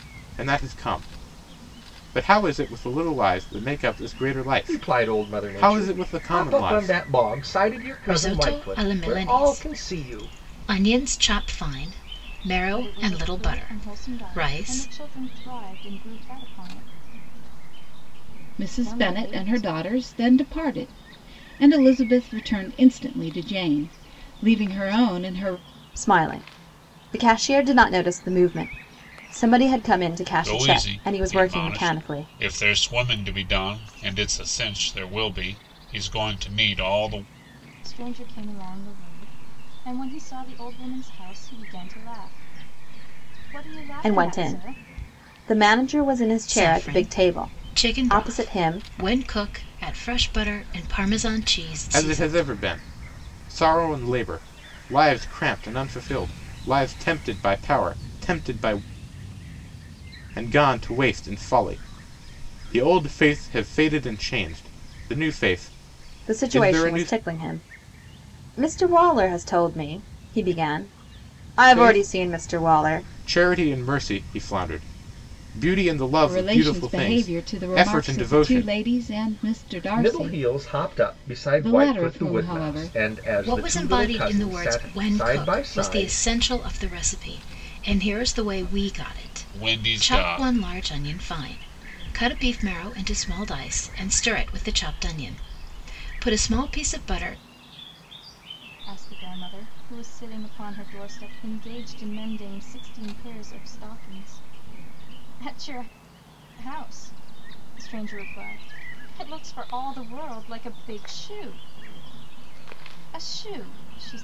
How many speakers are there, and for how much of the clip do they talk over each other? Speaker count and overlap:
7, about 22%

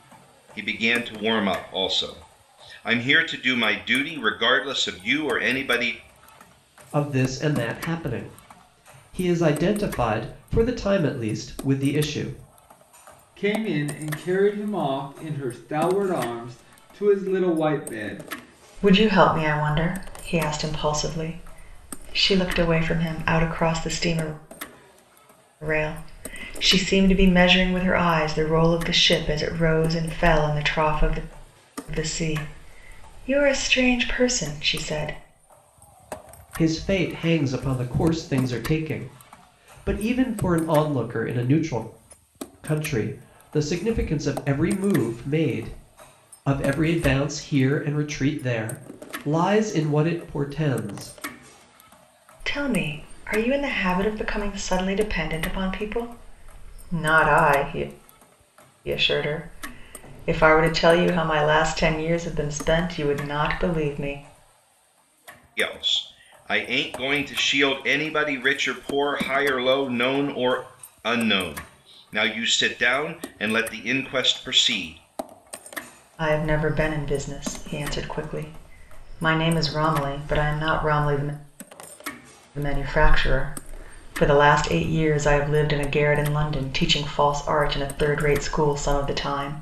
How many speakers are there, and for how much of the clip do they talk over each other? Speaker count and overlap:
4, no overlap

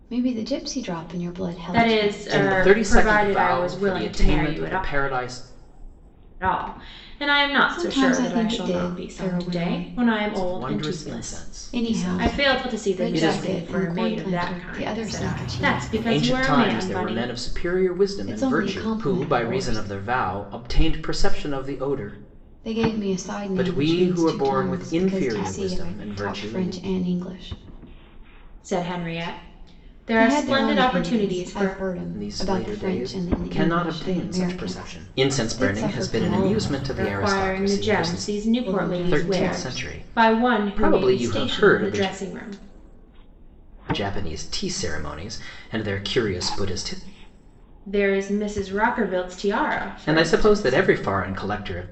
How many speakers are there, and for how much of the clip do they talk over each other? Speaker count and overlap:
3, about 56%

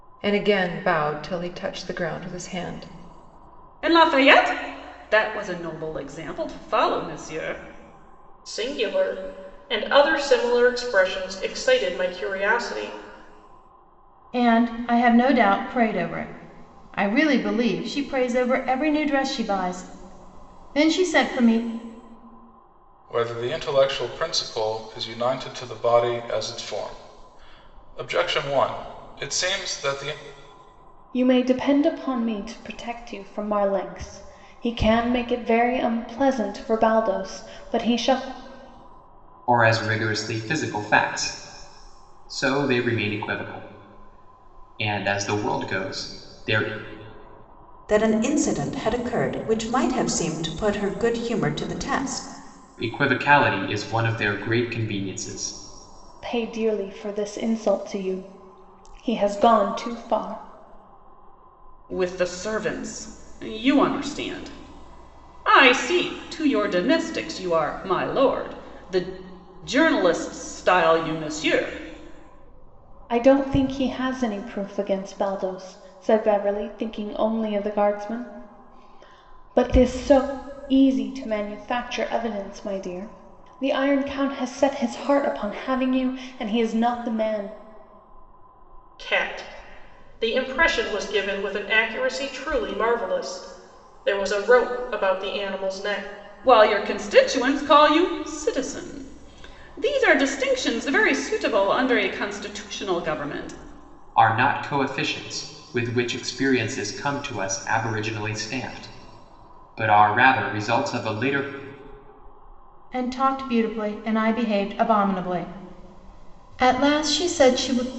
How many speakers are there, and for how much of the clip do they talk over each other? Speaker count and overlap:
8, no overlap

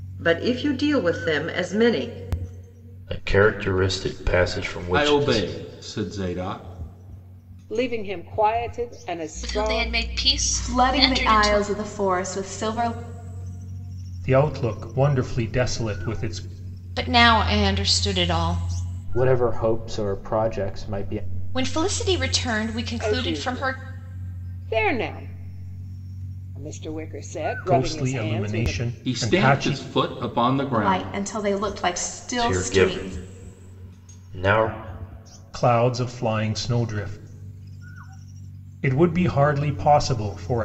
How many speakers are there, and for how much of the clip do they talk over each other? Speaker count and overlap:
9, about 16%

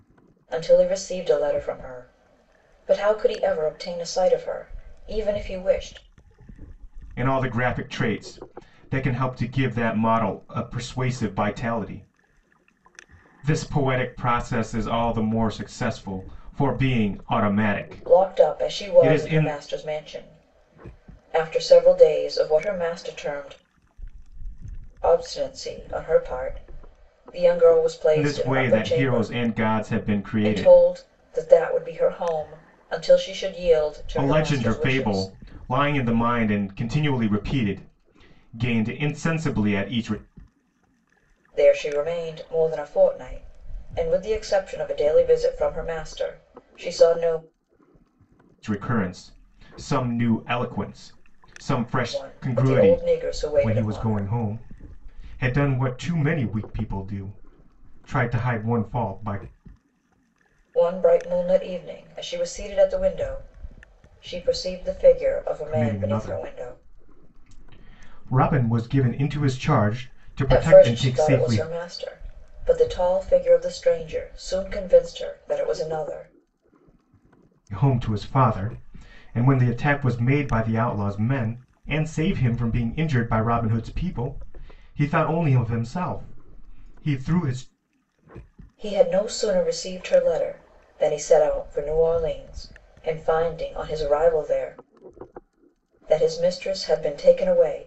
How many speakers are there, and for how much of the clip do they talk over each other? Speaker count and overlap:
2, about 8%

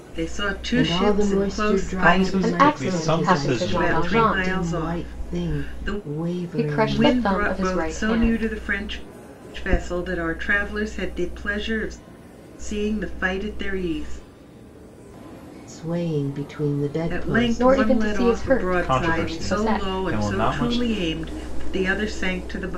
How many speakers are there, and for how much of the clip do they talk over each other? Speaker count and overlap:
4, about 49%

